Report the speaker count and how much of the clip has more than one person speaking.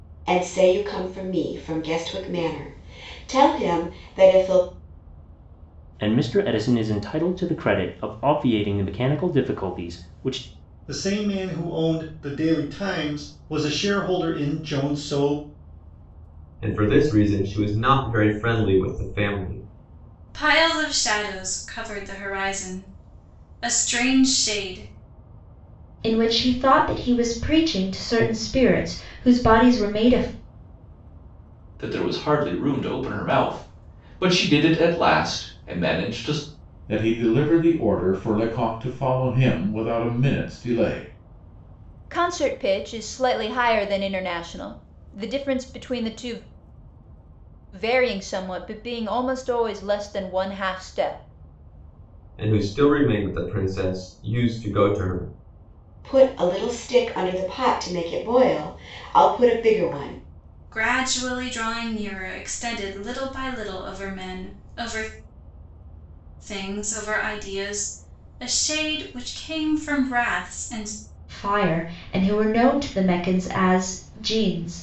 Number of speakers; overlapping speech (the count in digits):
9, no overlap